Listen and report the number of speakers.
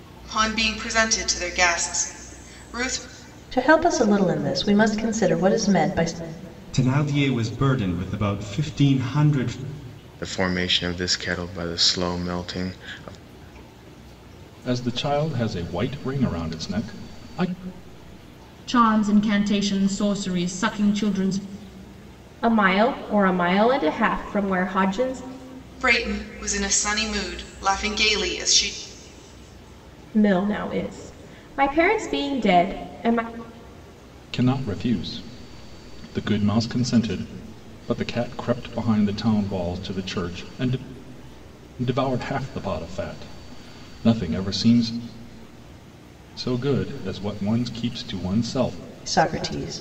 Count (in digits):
7